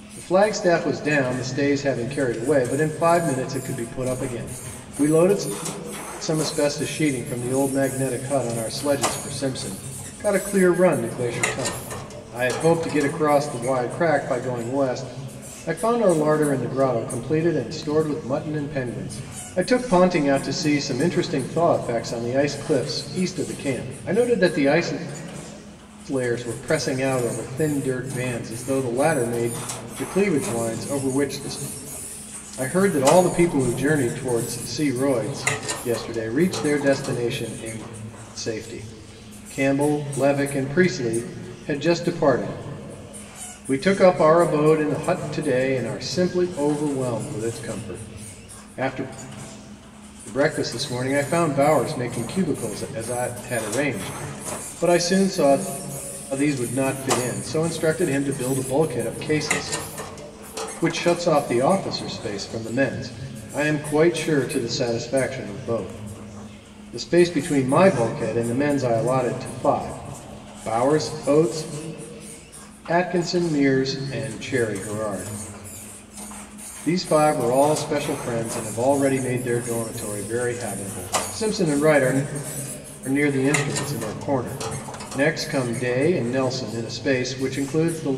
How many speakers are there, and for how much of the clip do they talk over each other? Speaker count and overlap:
one, no overlap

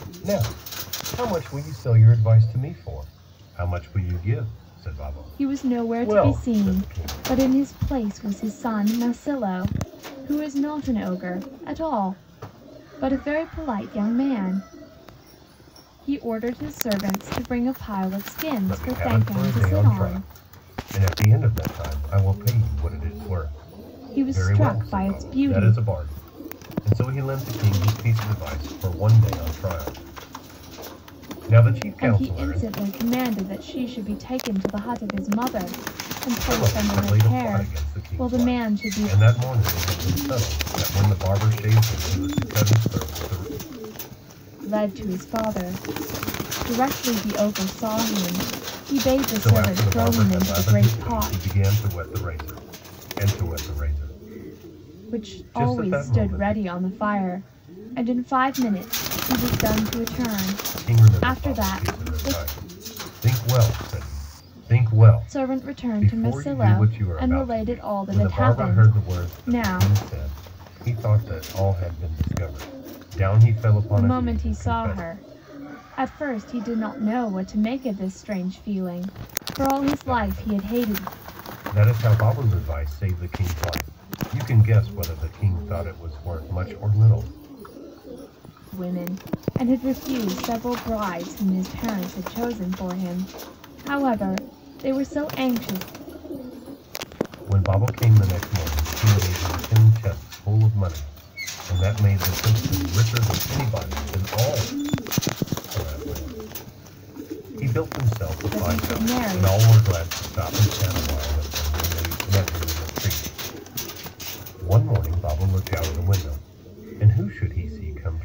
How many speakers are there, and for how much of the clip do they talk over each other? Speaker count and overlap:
two, about 19%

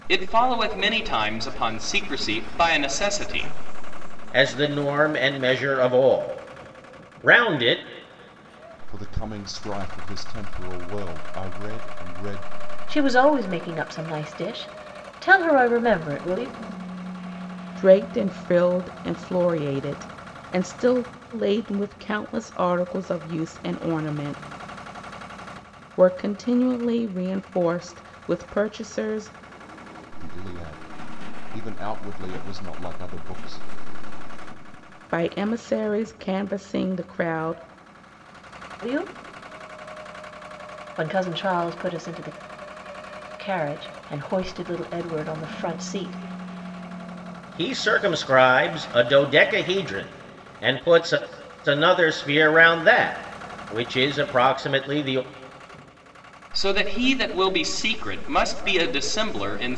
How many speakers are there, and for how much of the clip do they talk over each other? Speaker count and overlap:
five, no overlap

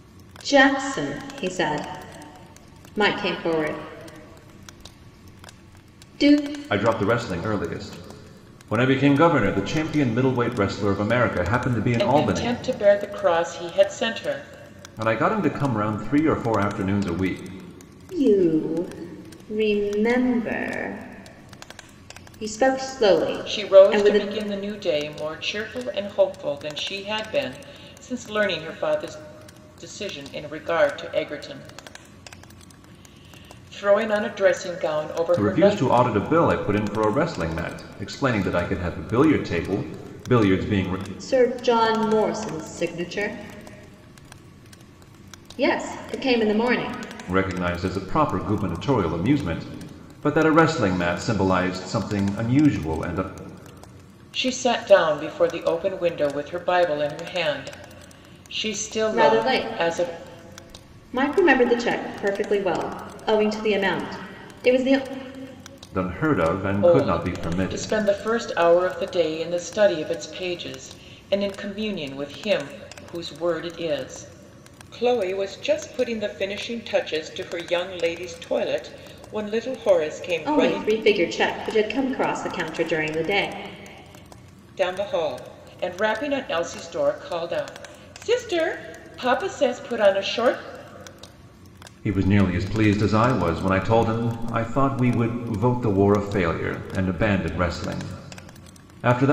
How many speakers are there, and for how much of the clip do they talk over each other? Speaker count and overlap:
three, about 5%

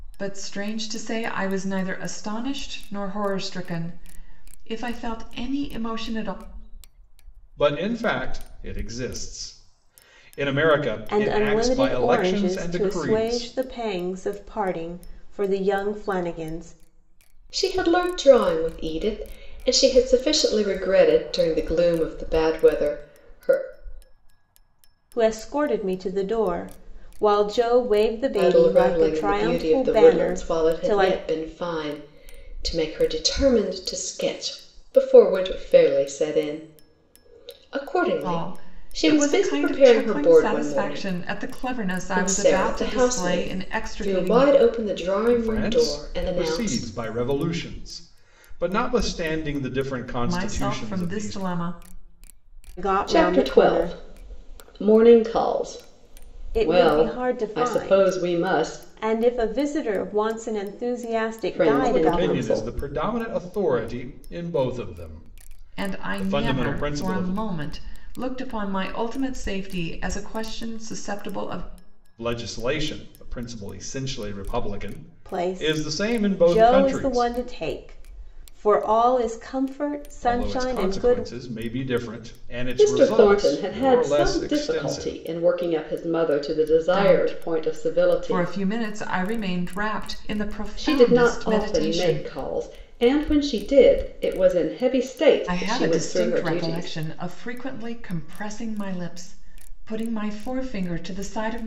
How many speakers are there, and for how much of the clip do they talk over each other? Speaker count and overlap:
four, about 29%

